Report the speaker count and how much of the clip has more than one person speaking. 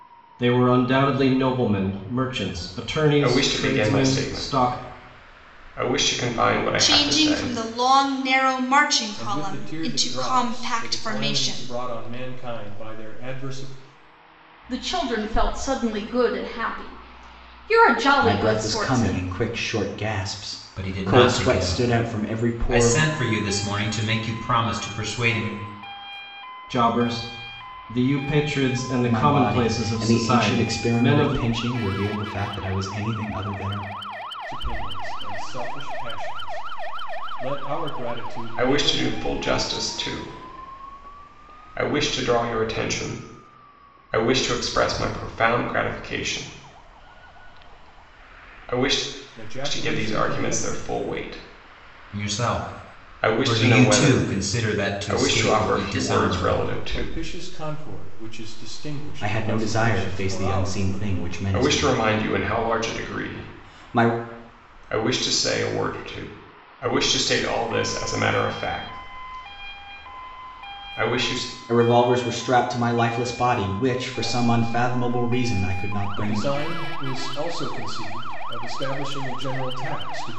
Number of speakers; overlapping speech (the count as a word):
seven, about 30%